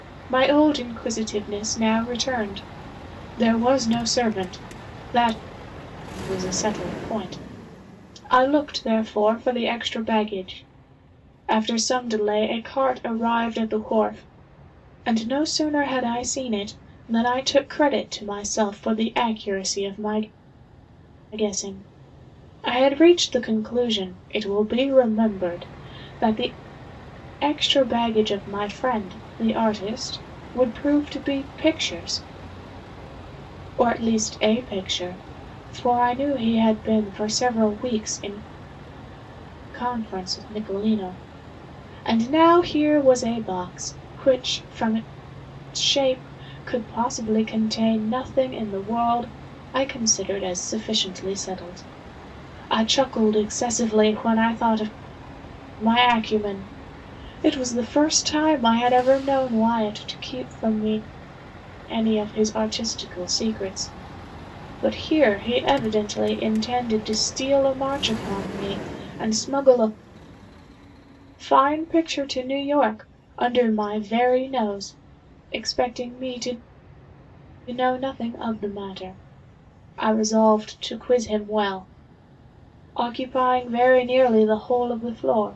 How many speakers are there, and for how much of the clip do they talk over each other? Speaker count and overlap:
1, no overlap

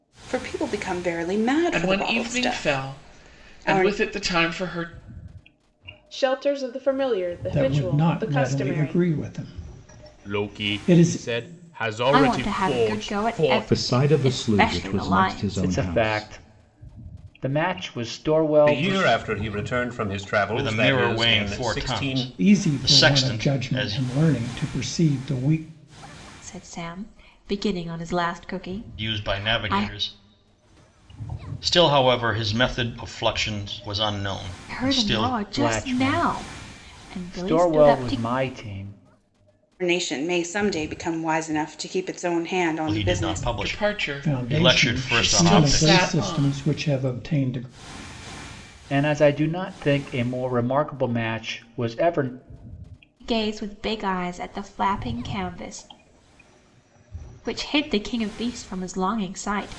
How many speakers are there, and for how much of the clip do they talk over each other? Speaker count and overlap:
10, about 35%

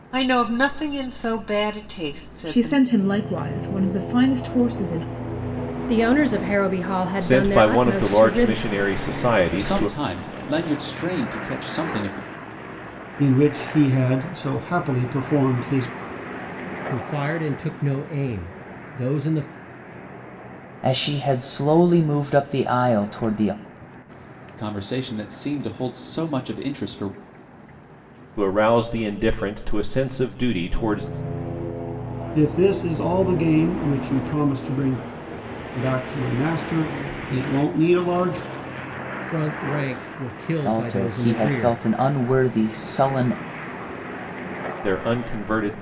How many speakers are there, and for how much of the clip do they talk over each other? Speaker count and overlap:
8, about 7%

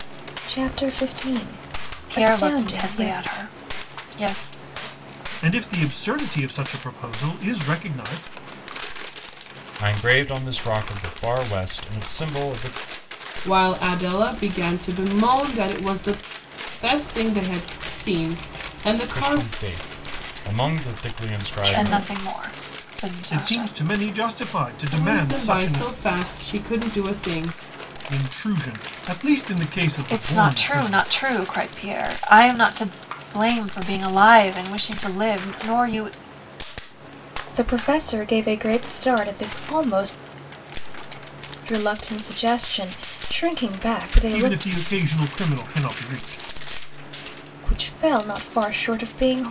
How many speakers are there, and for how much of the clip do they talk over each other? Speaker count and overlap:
5, about 10%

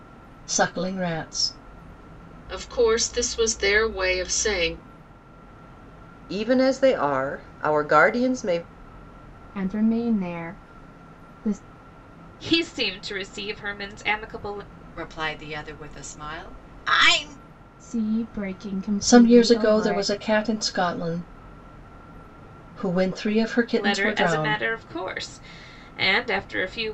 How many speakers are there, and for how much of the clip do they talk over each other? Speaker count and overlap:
6, about 8%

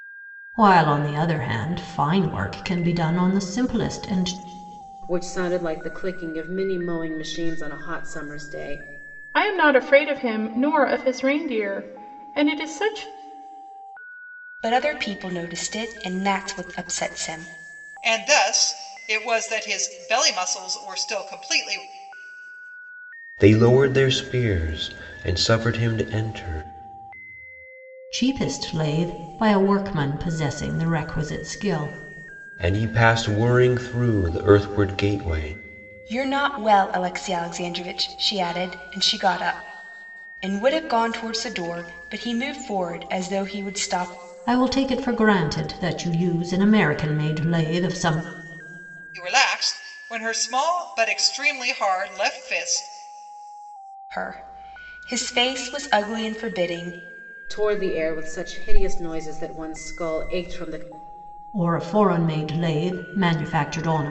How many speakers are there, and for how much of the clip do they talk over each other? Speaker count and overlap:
6, no overlap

